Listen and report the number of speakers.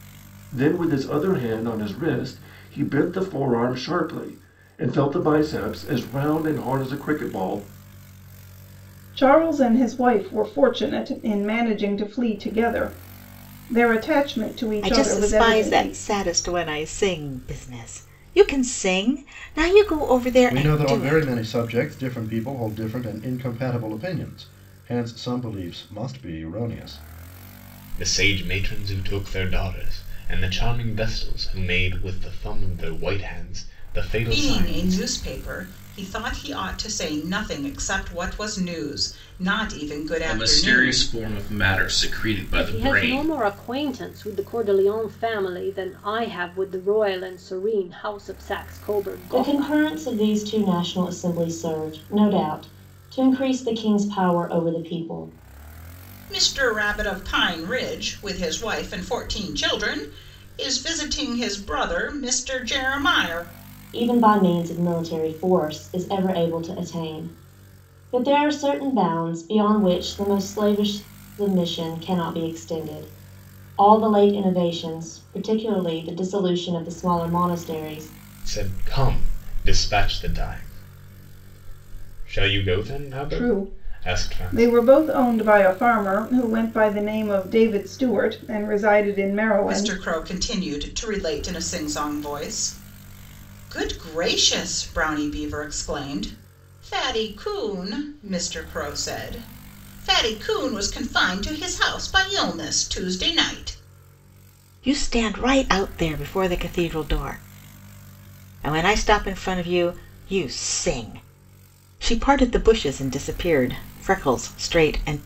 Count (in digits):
9